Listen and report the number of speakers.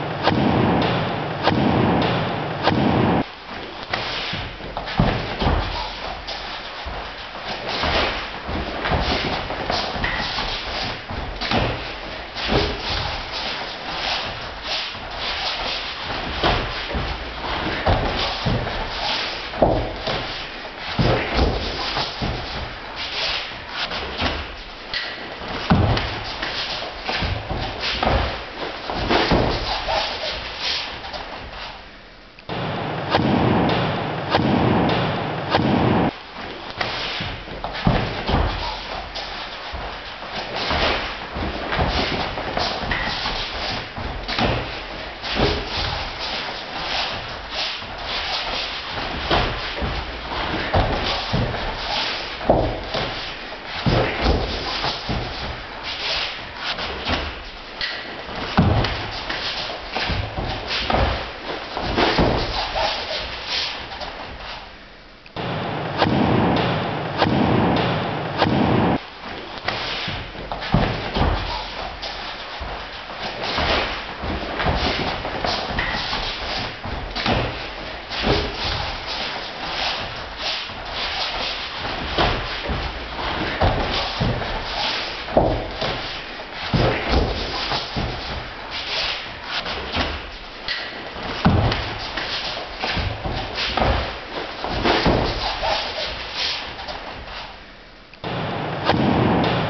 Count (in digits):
0